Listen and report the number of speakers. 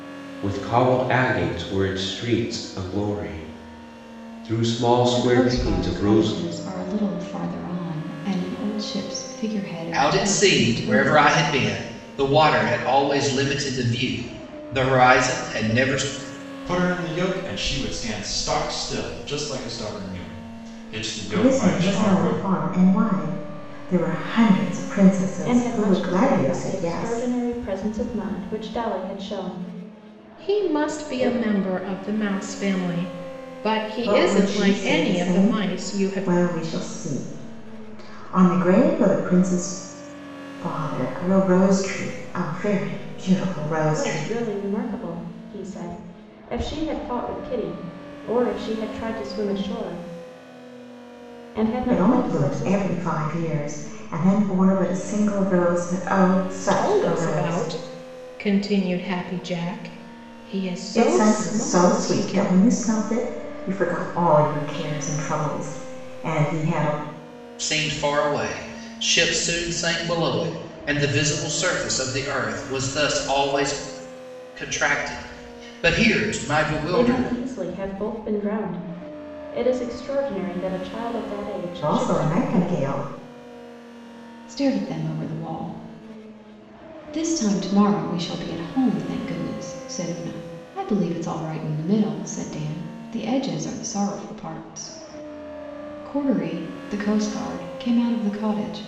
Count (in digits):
7